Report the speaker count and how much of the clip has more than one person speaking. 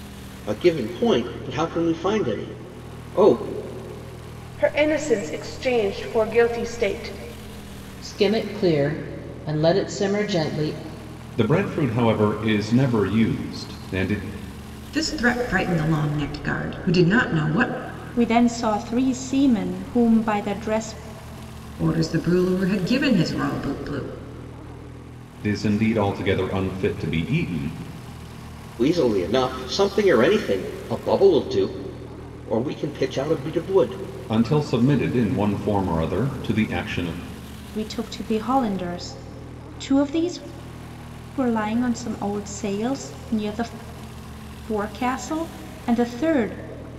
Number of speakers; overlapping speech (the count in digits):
6, no overlap